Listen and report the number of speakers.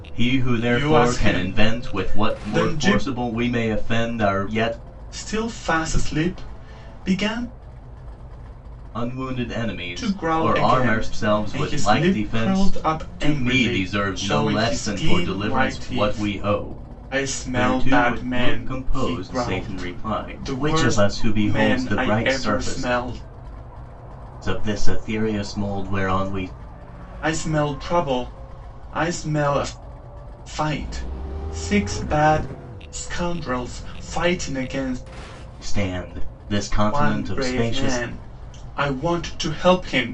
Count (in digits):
2